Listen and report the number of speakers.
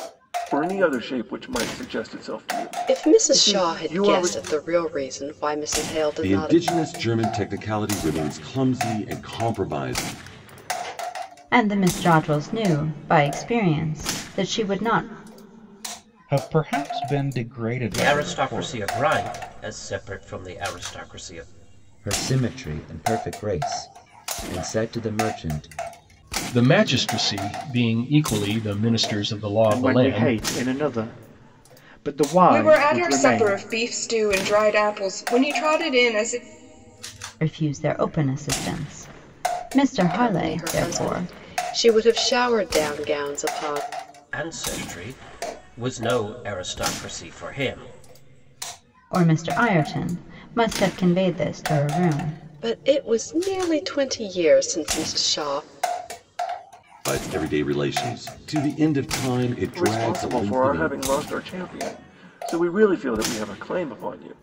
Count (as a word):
ten